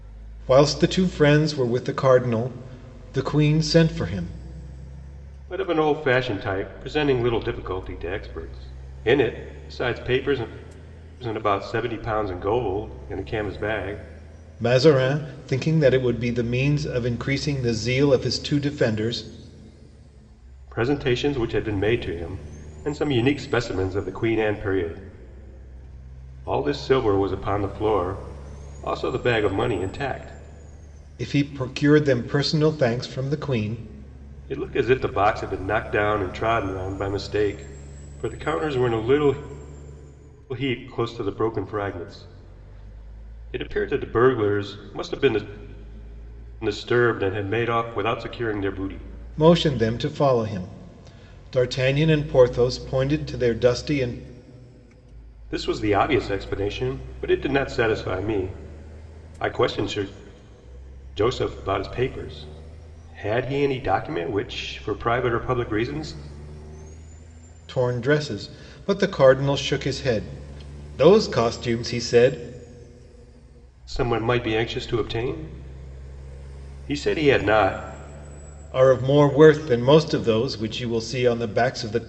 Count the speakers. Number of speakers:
2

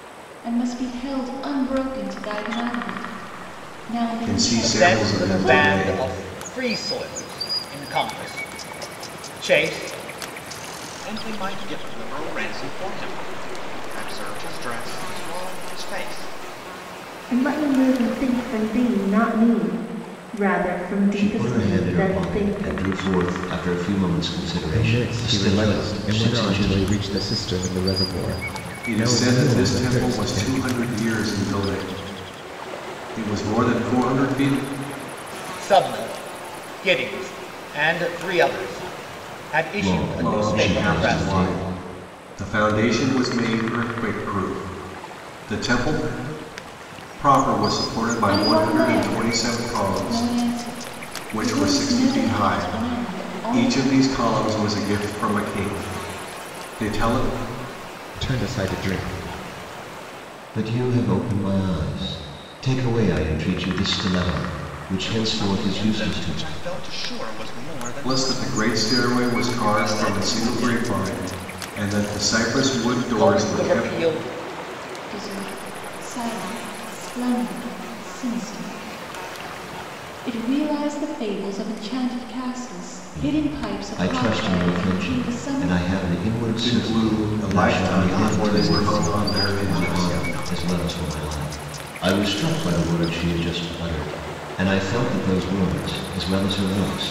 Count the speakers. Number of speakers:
7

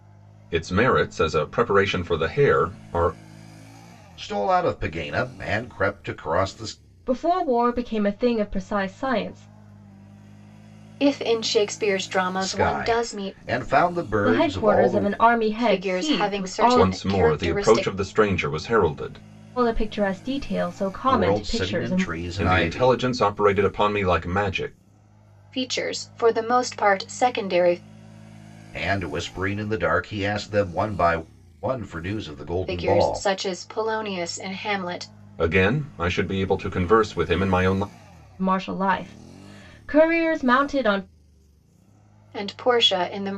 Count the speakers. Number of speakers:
4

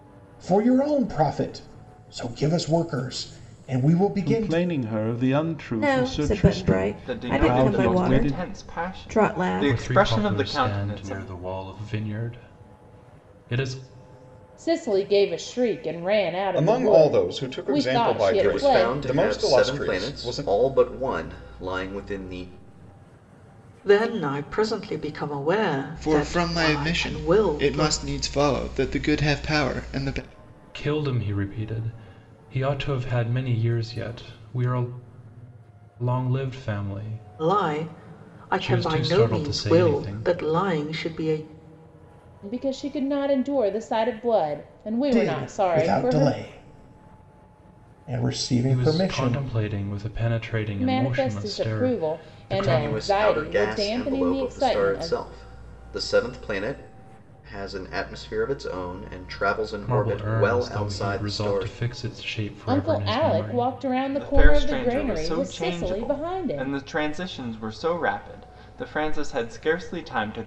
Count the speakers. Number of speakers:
10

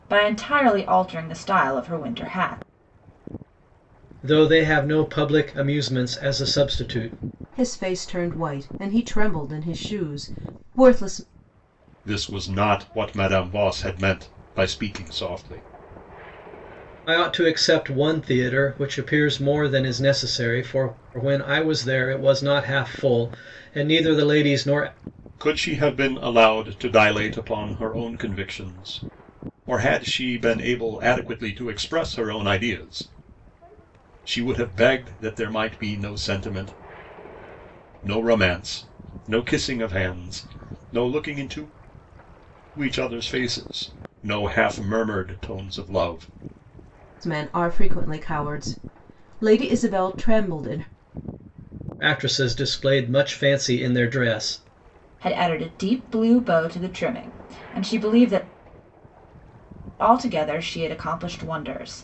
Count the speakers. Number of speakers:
4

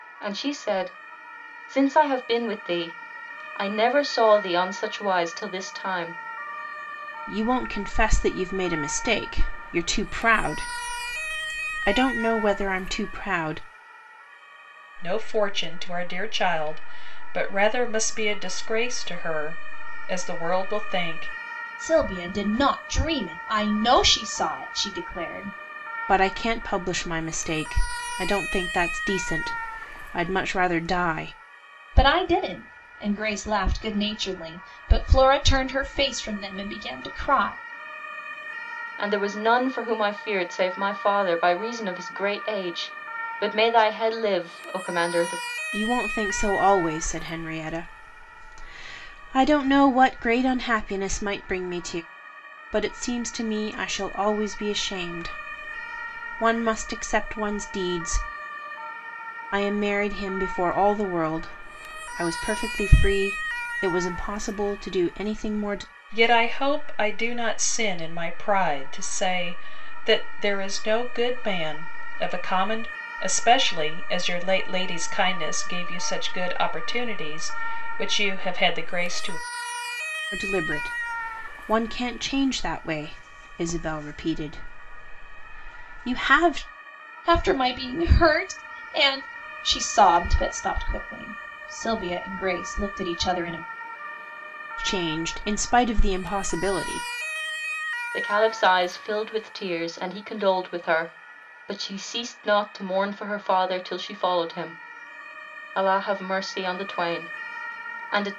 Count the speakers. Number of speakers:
4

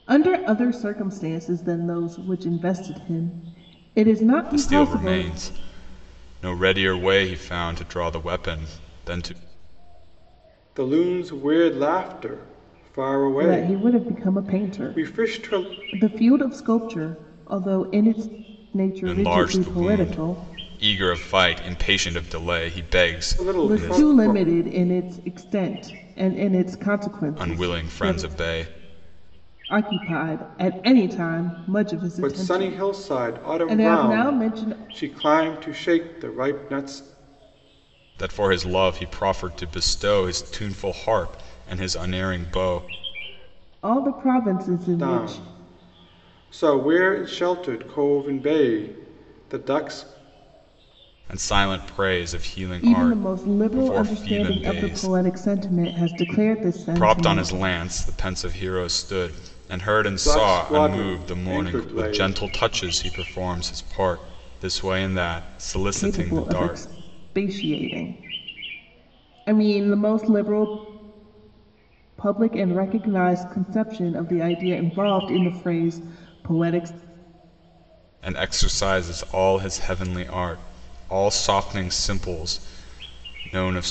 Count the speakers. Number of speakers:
3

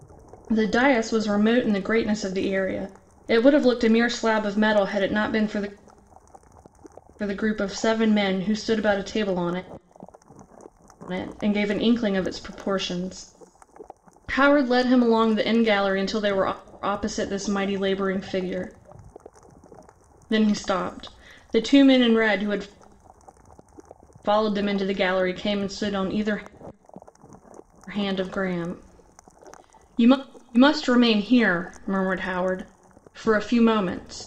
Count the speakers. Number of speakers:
1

